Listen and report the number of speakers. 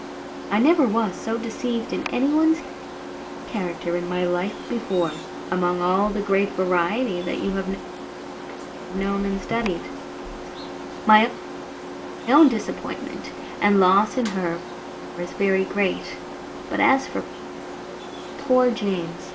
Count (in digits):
1